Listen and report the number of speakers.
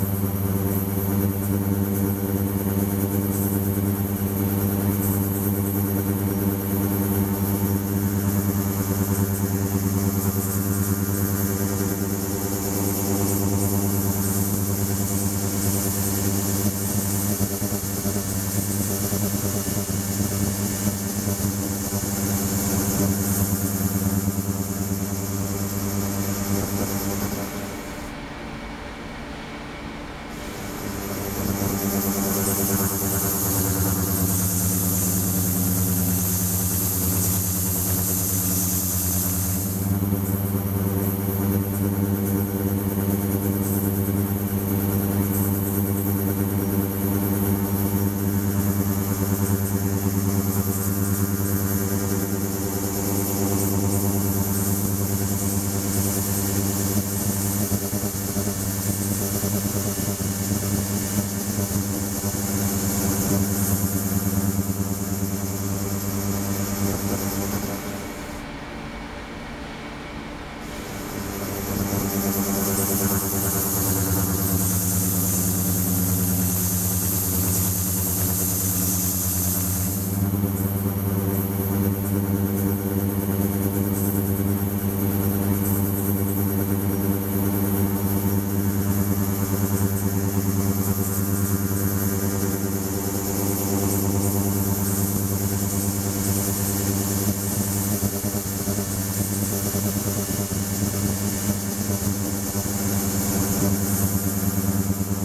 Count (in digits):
0